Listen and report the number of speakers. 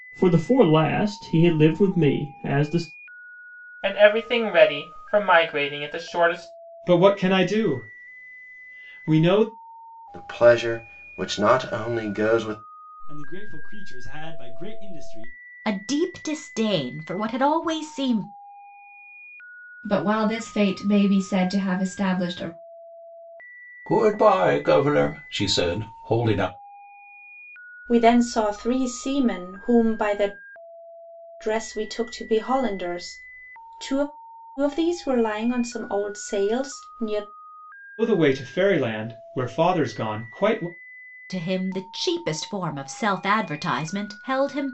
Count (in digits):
9